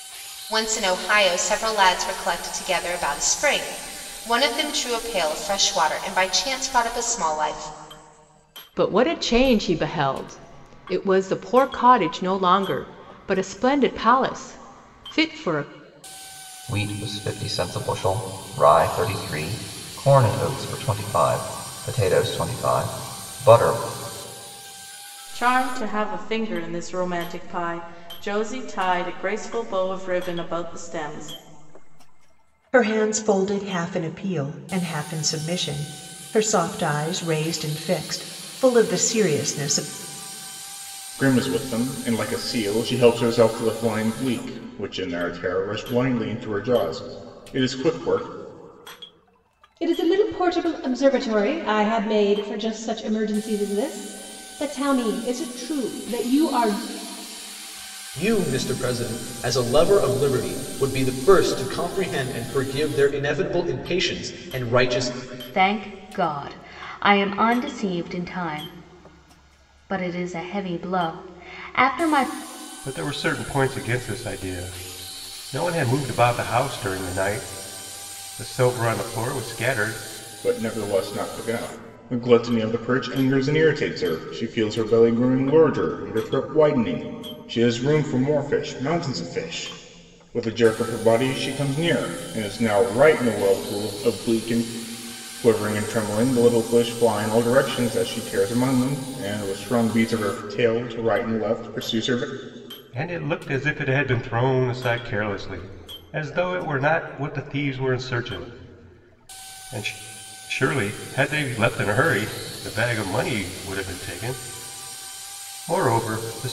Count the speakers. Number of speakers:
10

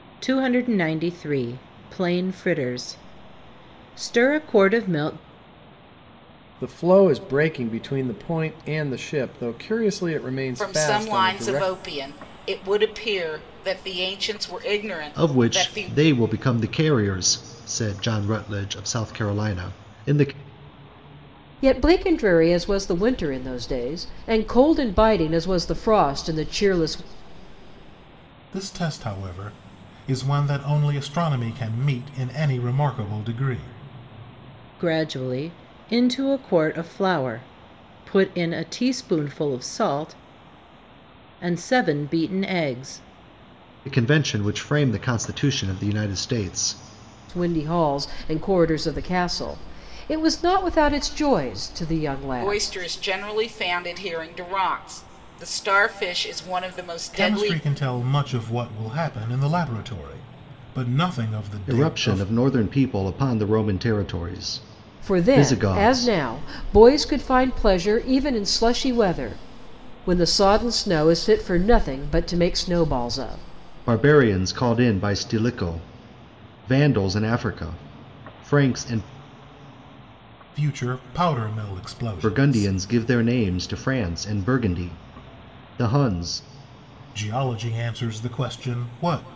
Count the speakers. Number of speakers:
6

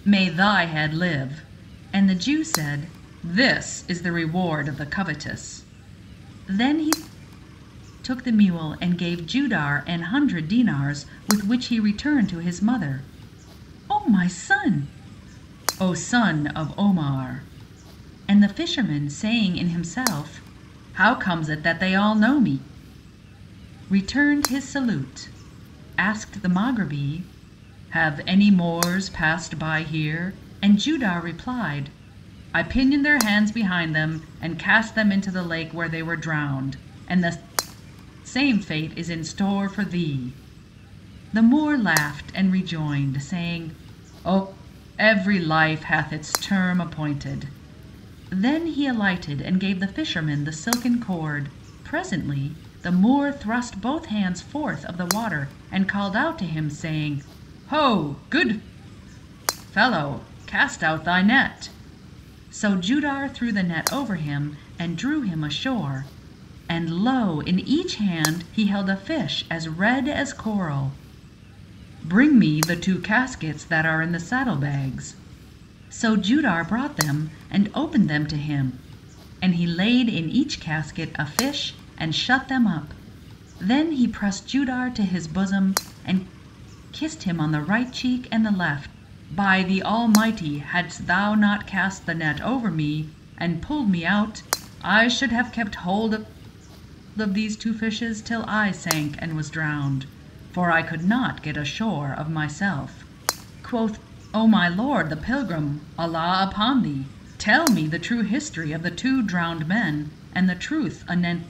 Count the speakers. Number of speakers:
1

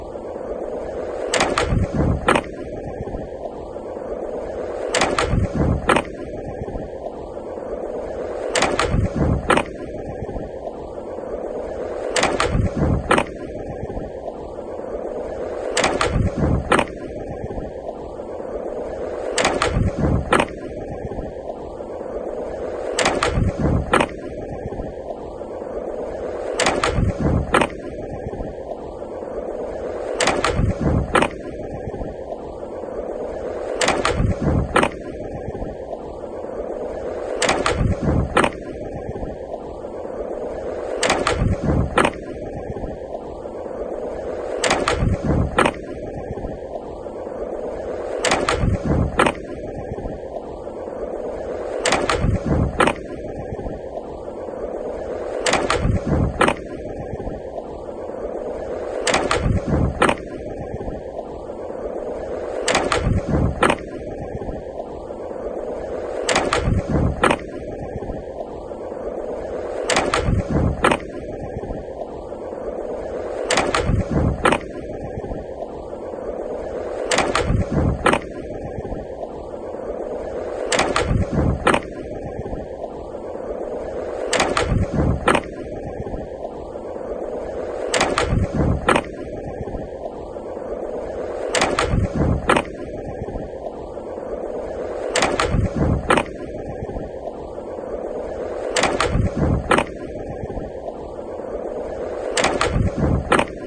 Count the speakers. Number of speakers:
0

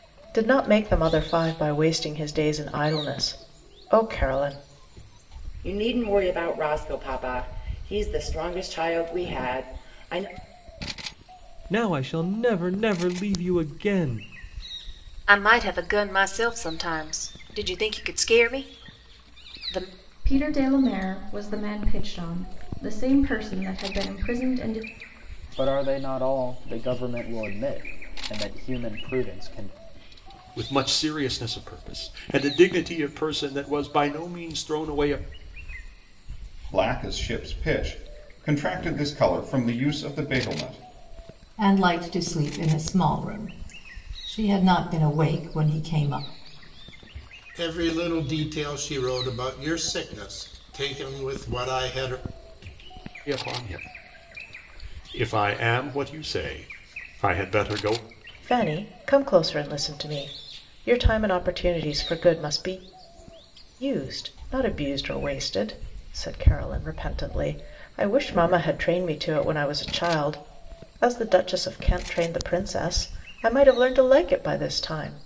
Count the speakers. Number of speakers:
10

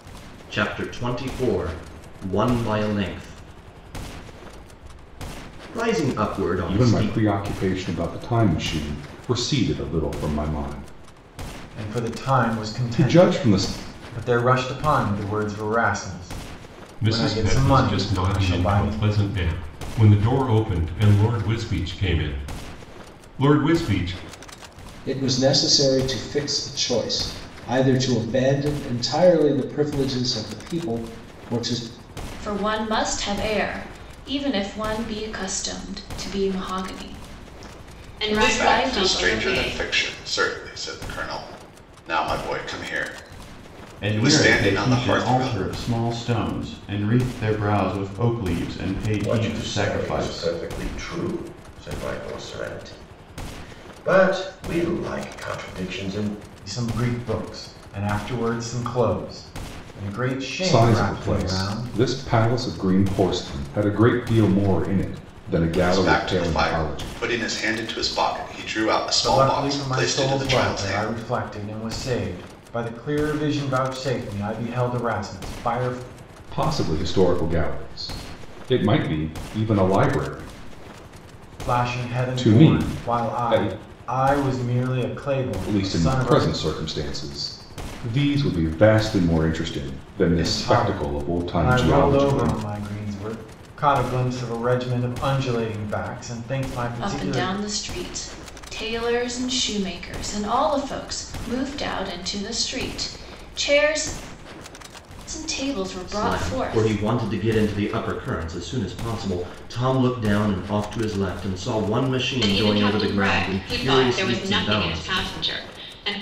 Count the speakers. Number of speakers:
10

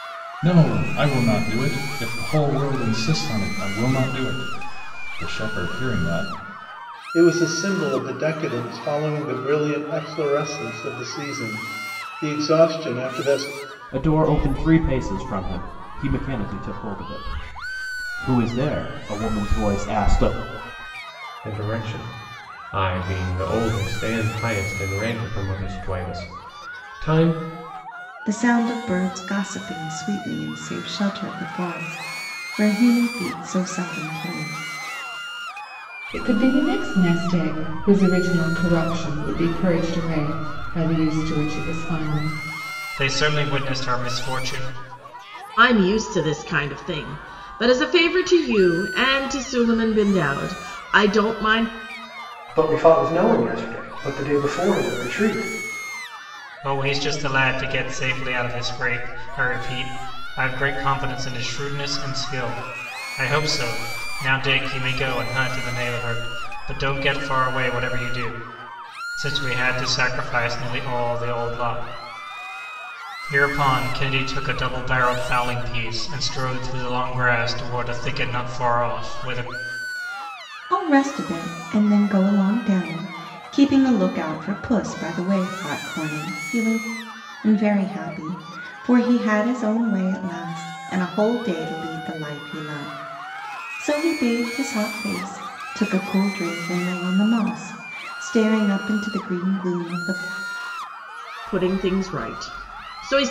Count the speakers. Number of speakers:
9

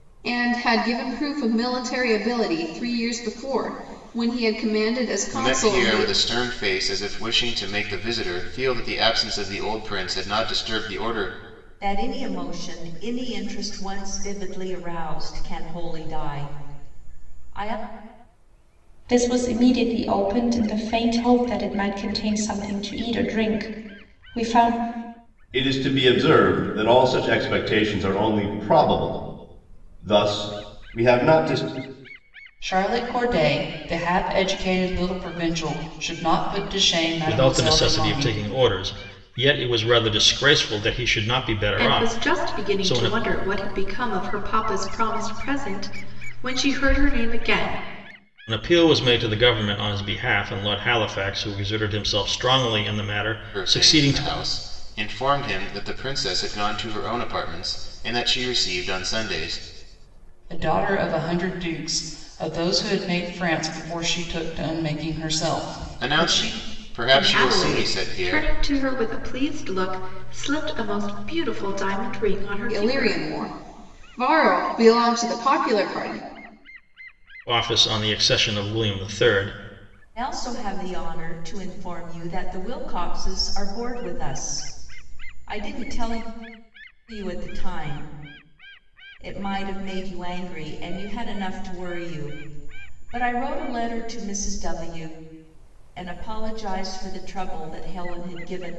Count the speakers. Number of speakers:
8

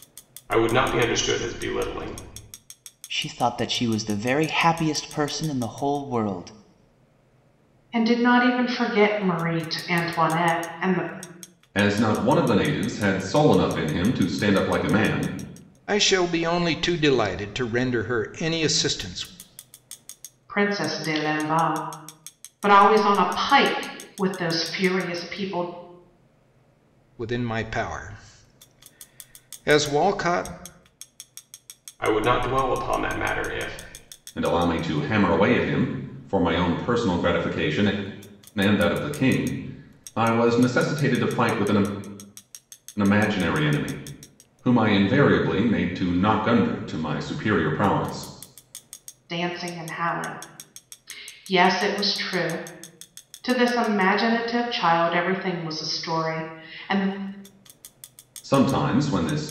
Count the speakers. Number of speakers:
5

